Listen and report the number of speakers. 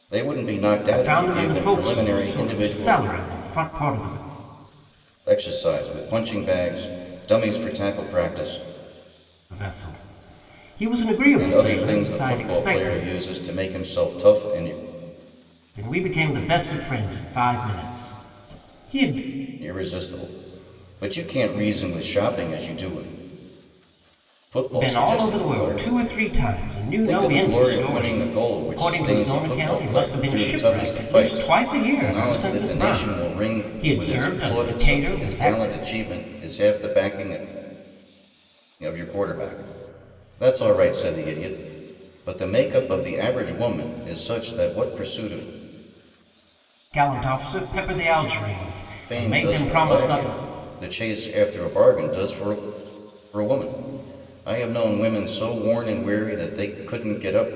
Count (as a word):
two